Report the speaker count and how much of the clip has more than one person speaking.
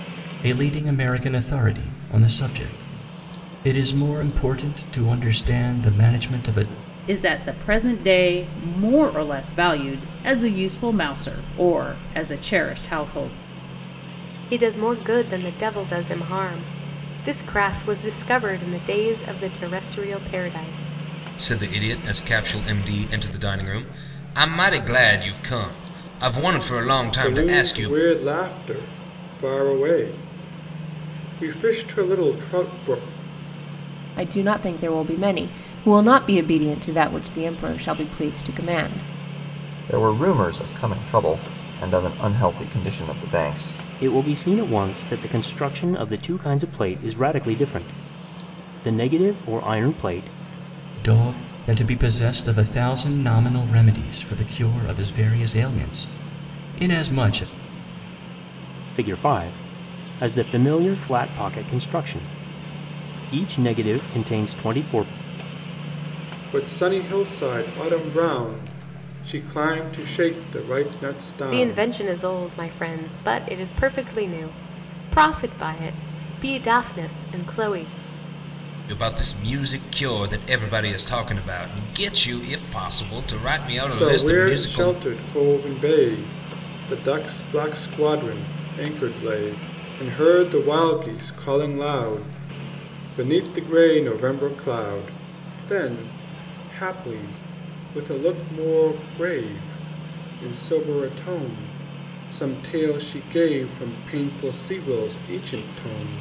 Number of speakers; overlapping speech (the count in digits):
8, about 2%